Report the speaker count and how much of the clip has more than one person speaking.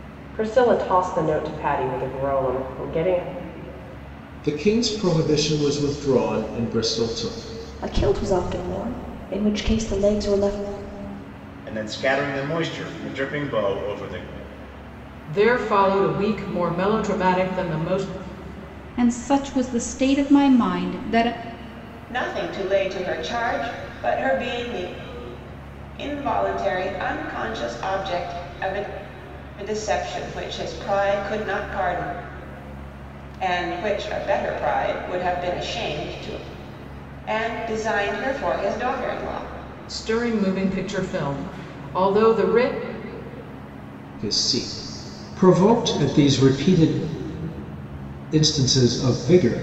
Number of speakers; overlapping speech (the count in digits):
7, no overlap